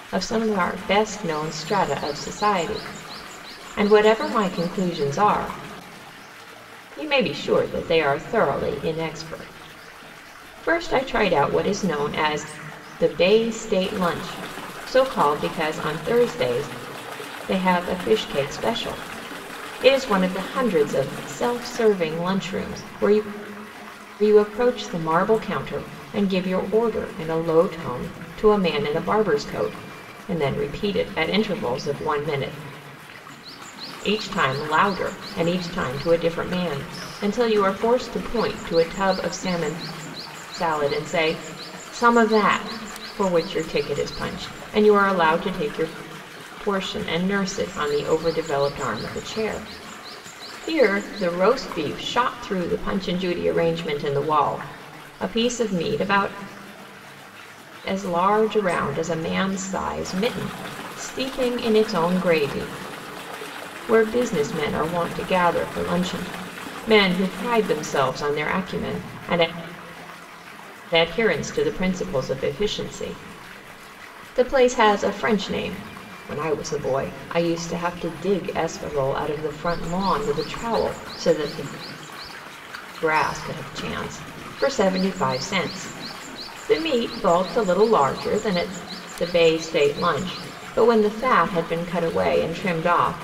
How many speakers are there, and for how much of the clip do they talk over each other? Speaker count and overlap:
one, no overlap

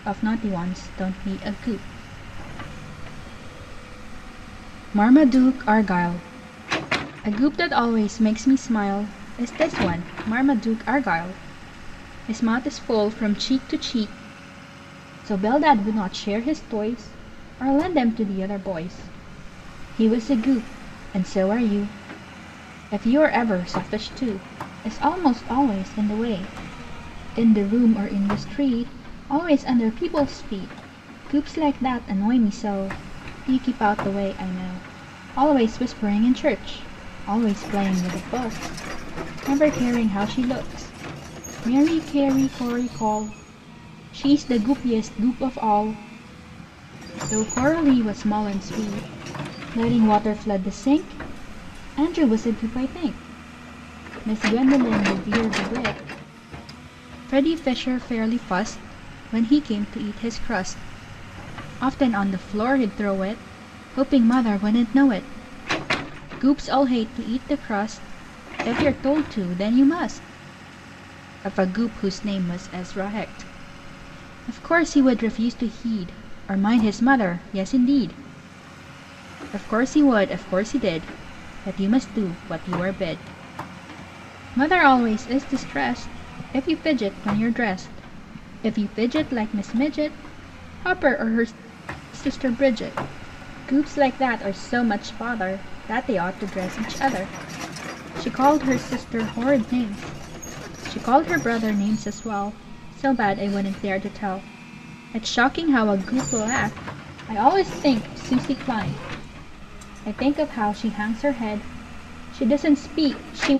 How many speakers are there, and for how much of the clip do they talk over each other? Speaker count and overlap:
one, no overlap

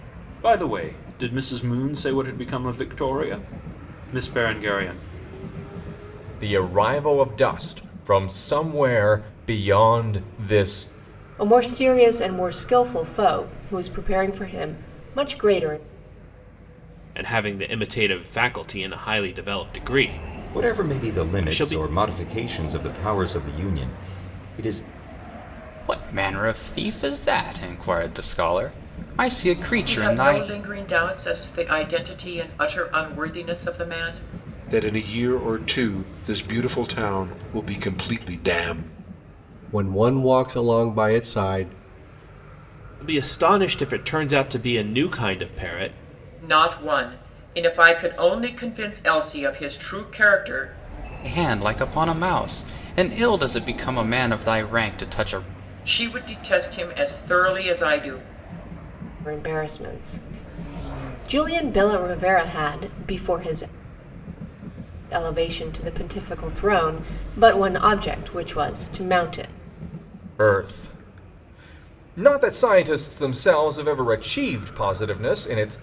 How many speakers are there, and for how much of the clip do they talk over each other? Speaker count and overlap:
nine, about 3%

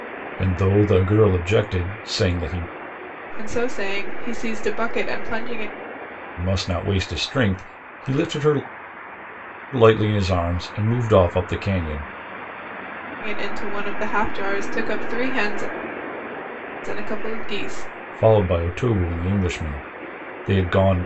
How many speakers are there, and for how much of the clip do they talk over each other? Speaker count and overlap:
two, no overlap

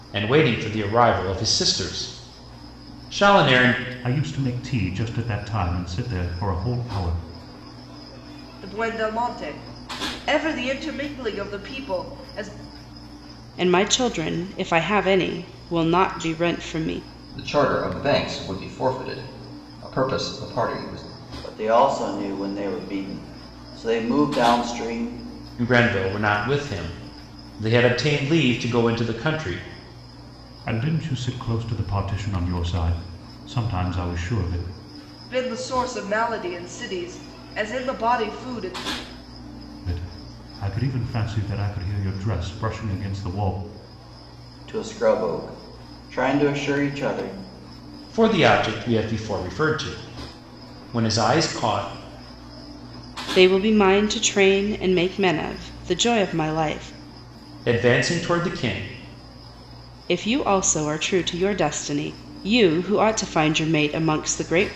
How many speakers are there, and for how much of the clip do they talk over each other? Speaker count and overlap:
six, no overlap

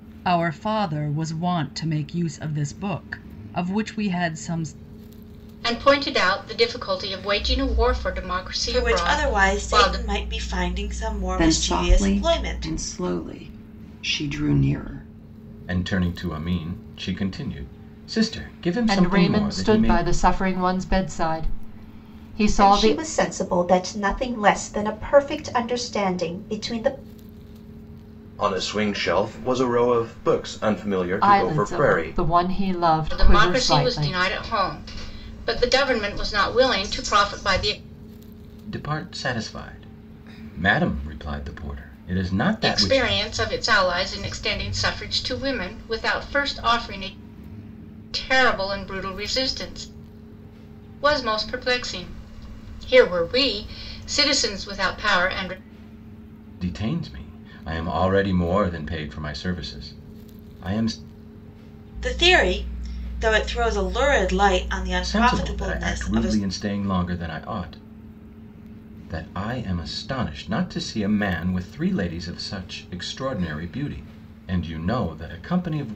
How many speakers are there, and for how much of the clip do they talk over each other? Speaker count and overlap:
eight, about 11%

